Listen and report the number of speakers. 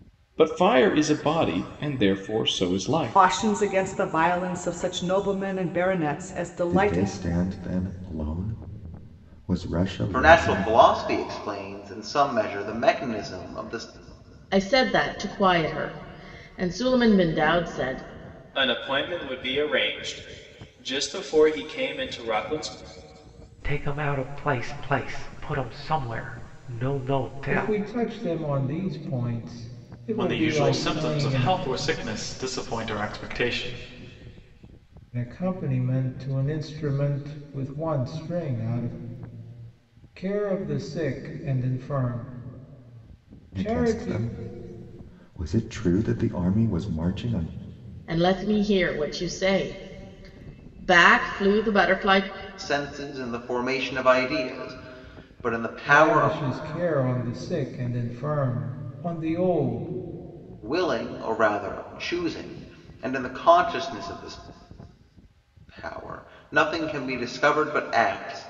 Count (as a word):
nine